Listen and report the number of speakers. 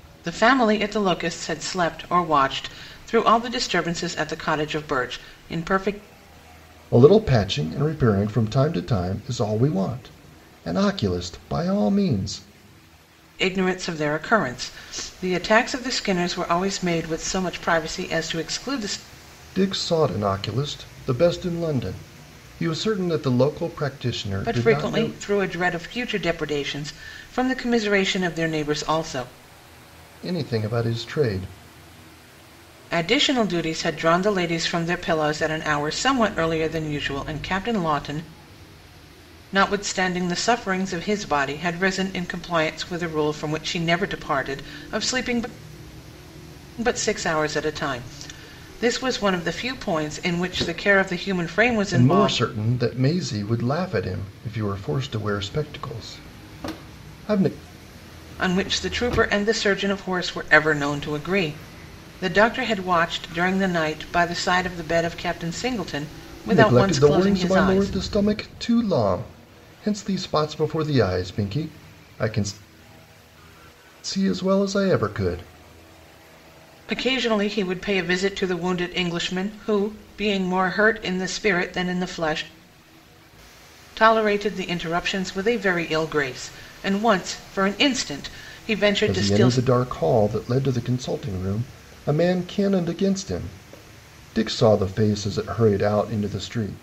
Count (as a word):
two